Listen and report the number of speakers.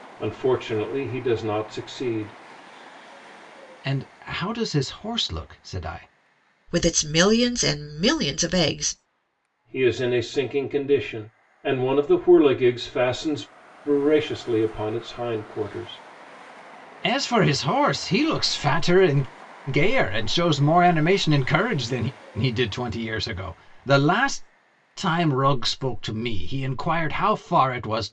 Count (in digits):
3